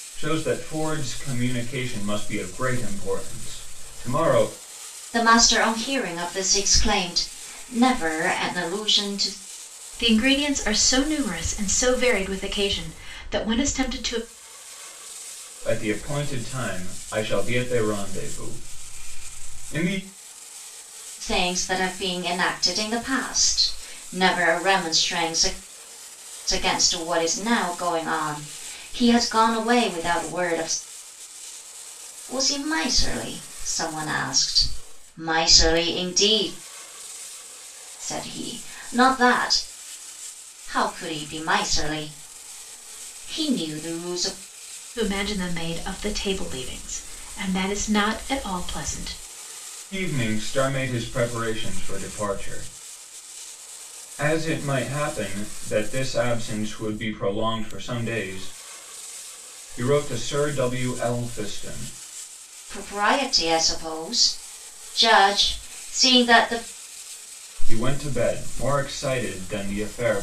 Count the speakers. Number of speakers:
three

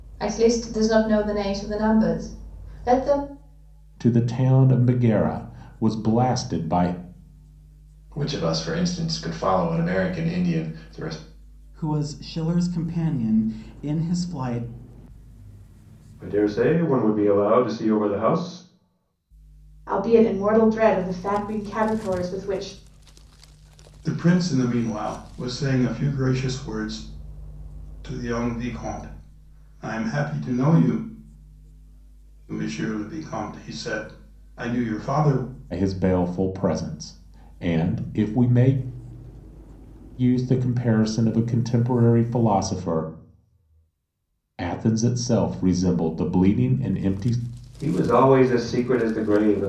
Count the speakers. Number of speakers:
seven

